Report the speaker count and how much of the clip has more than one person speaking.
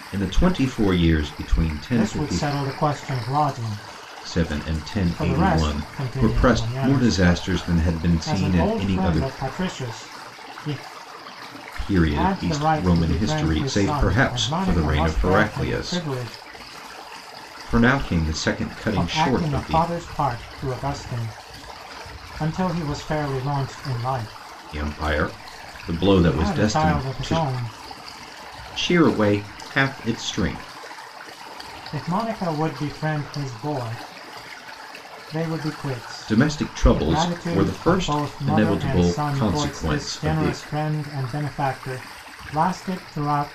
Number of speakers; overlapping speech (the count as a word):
two, about 32%